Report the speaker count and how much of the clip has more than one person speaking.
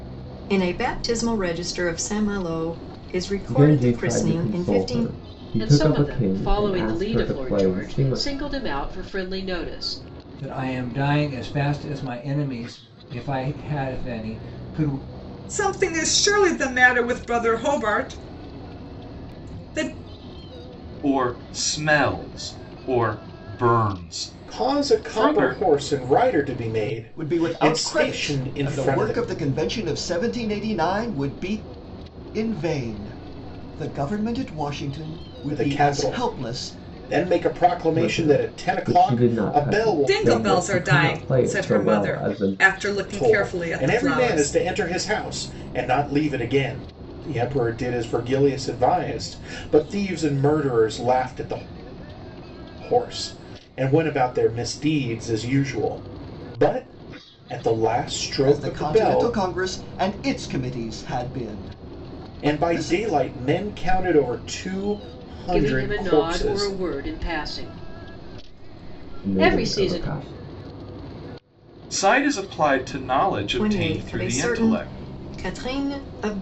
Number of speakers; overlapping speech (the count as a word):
eight, about 26%